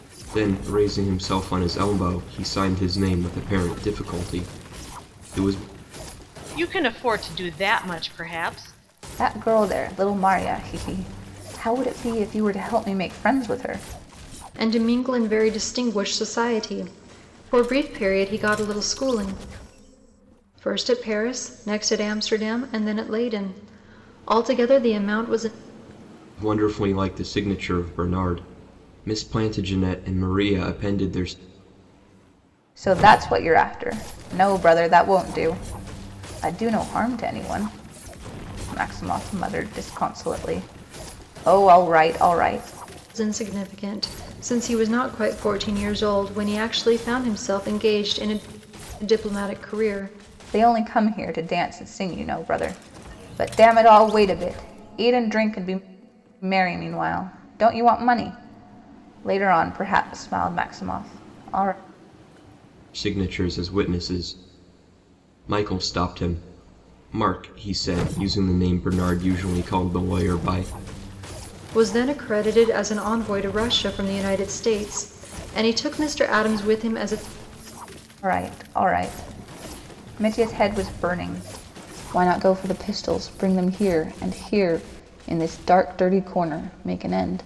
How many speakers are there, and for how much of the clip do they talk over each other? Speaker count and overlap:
four, no overlap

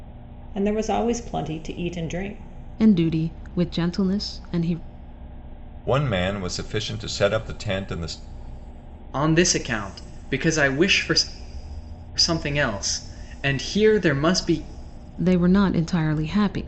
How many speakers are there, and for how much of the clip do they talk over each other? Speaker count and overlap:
four, no overlap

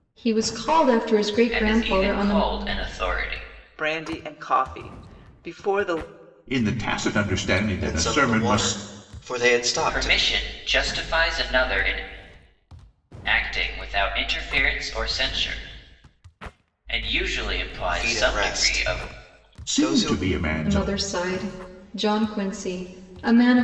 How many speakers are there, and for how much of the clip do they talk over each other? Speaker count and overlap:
five, about 19%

